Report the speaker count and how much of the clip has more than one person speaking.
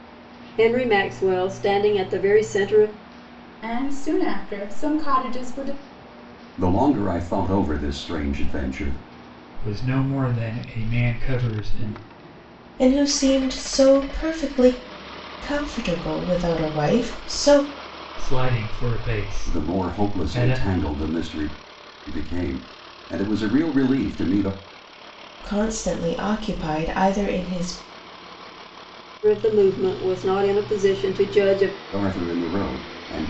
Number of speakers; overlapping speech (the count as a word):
five, about 3%